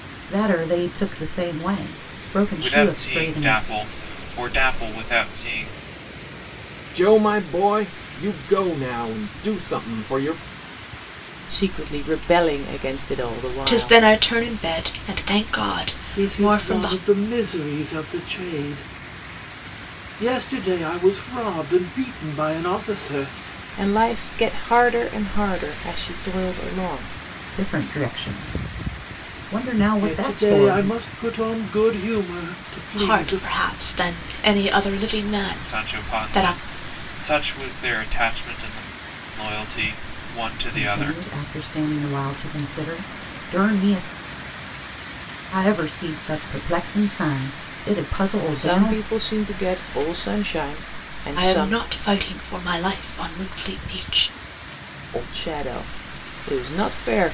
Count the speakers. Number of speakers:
6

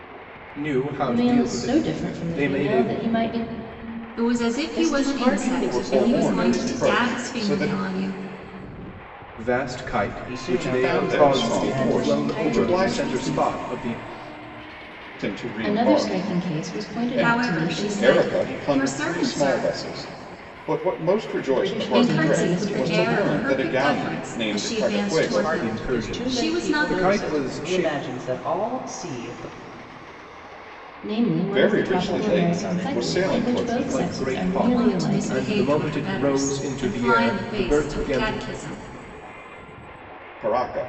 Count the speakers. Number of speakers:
5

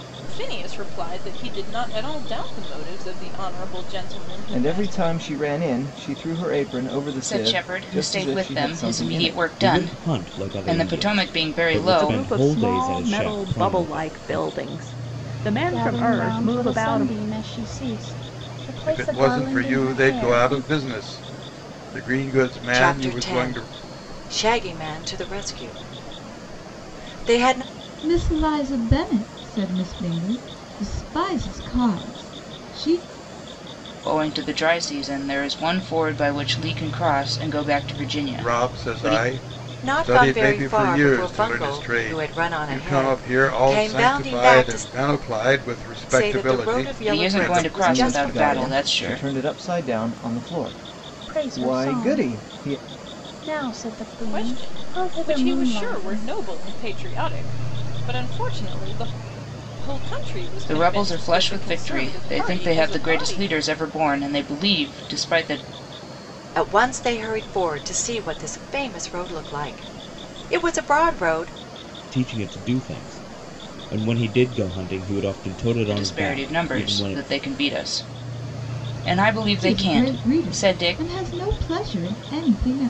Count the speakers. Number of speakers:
9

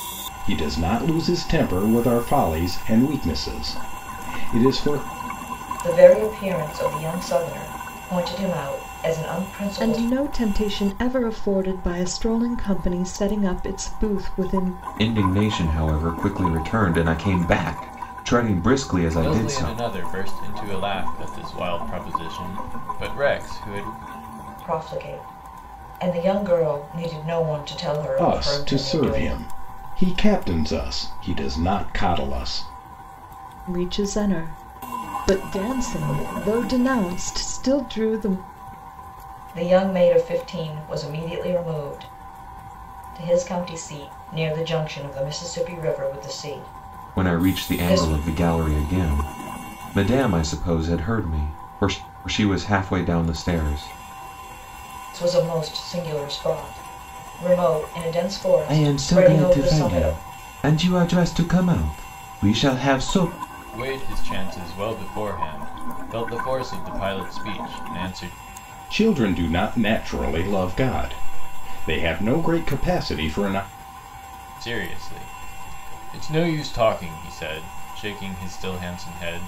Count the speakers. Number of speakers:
5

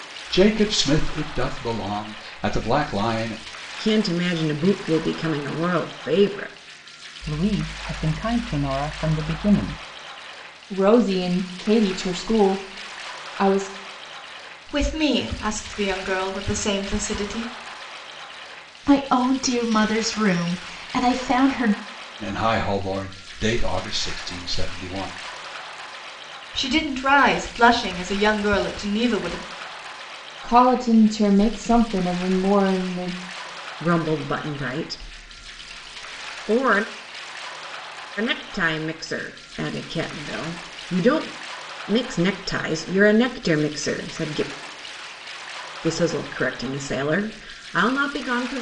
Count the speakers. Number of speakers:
6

